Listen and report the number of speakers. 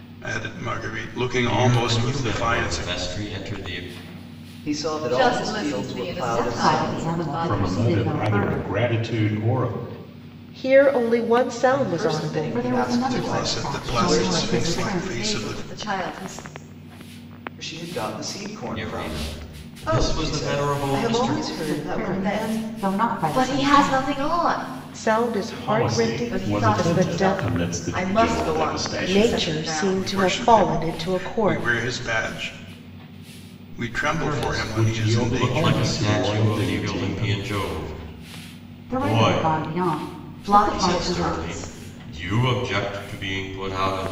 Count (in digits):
7